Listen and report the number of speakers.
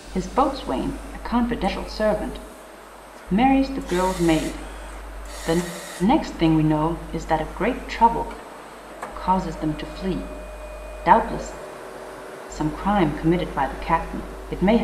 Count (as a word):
one